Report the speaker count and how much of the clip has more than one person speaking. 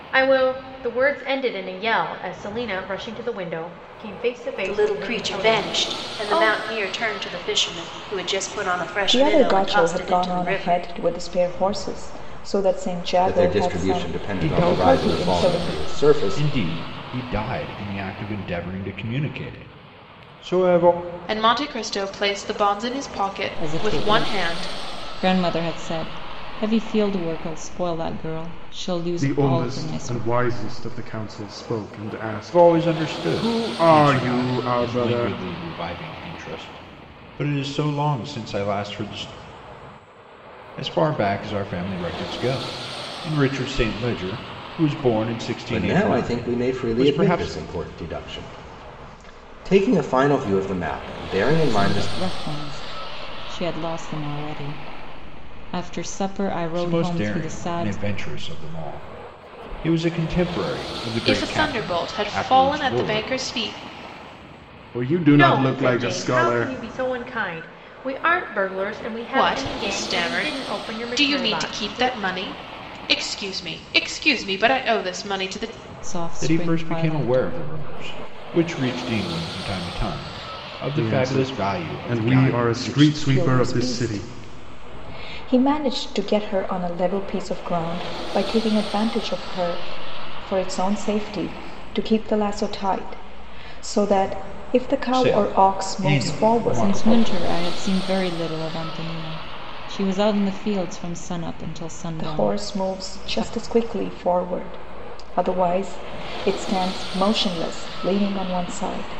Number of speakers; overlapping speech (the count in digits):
8, about 28%